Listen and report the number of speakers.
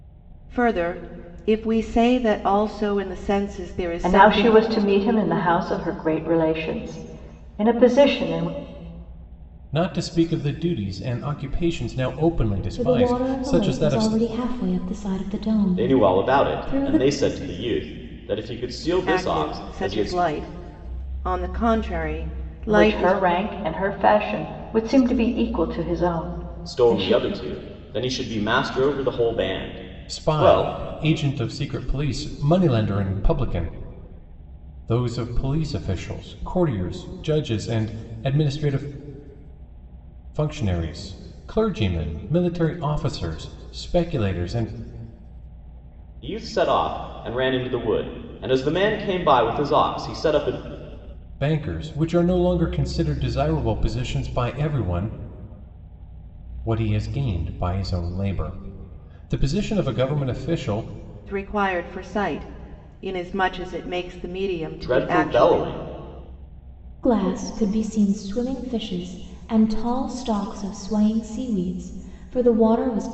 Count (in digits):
5